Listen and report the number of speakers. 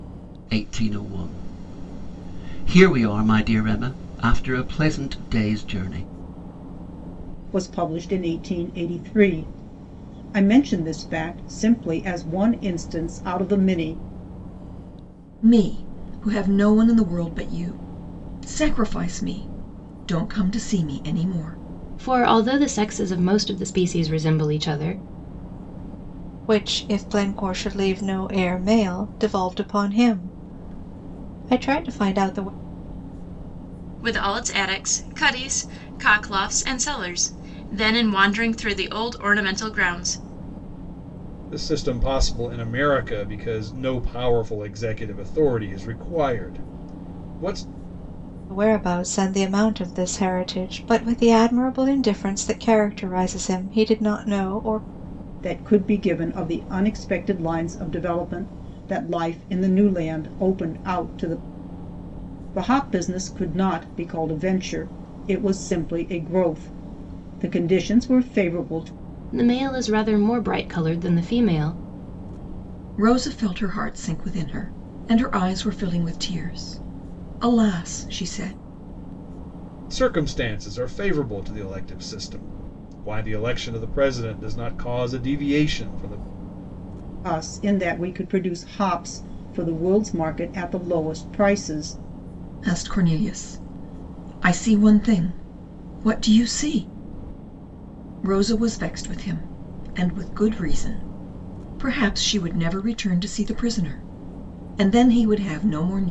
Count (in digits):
7